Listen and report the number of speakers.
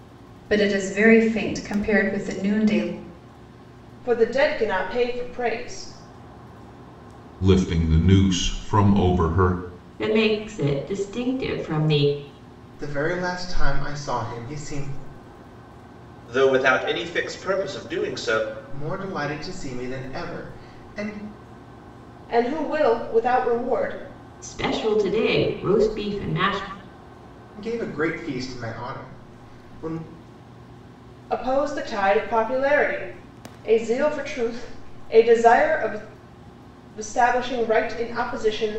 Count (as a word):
six